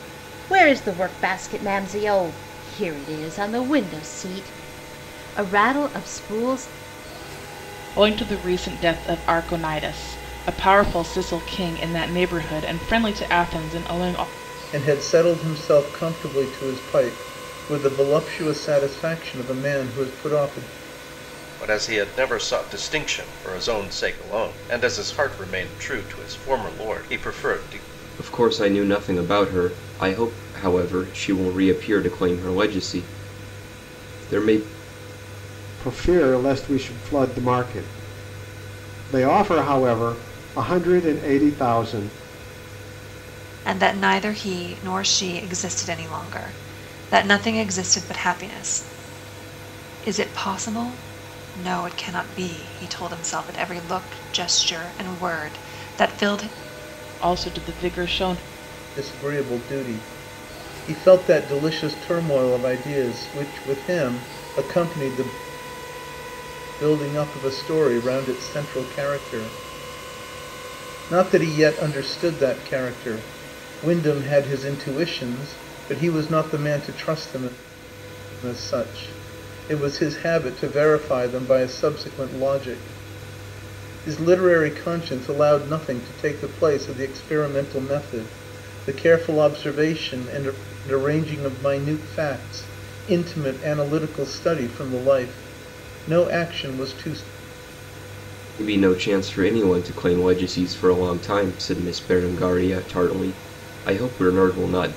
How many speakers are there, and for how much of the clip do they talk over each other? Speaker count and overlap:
7, no overlap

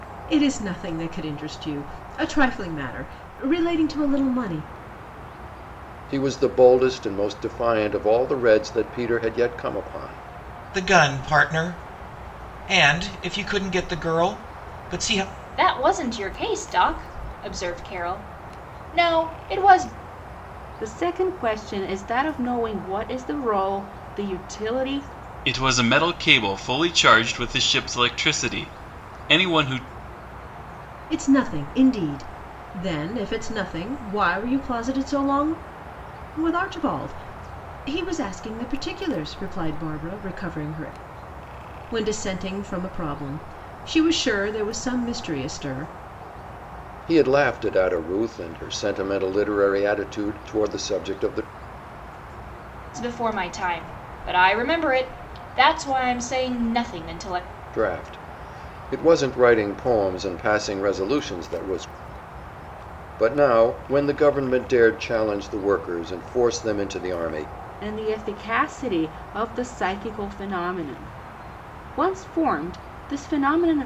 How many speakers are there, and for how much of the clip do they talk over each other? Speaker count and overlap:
6, no overlap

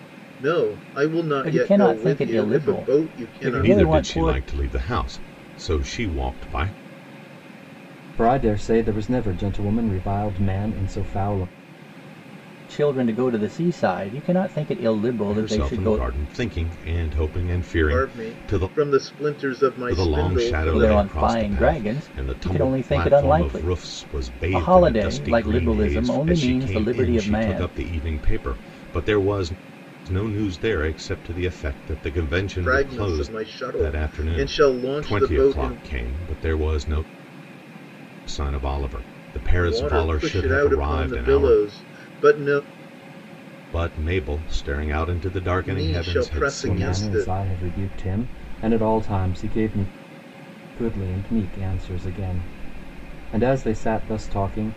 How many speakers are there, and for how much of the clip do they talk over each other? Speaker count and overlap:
4, about 33%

